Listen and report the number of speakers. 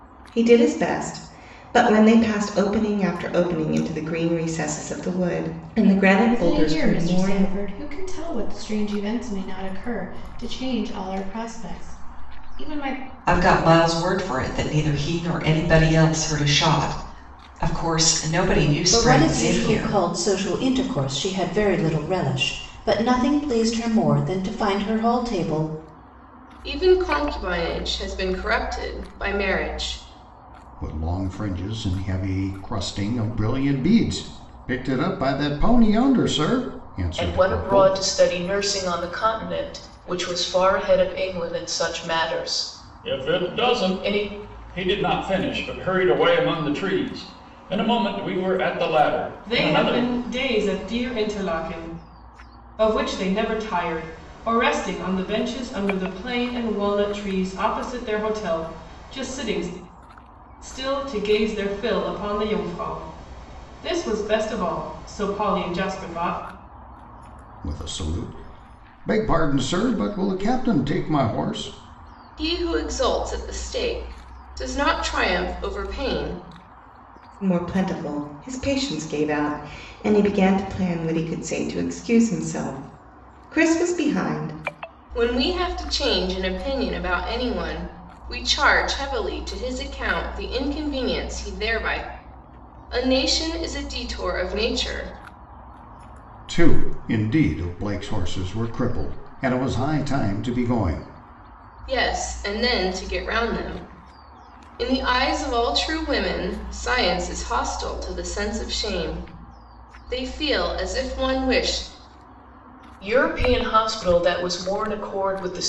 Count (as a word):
nine